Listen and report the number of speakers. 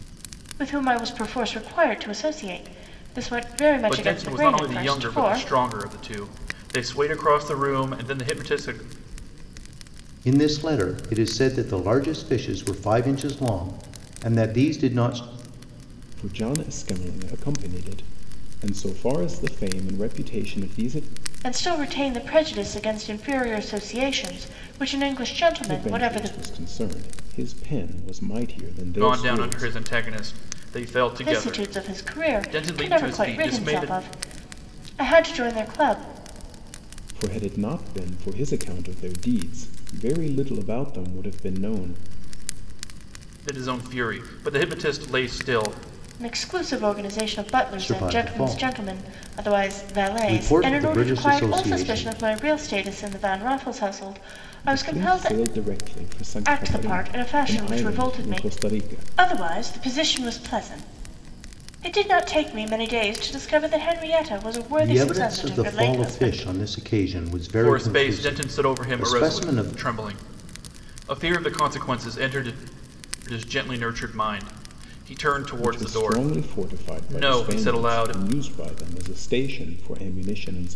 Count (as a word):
four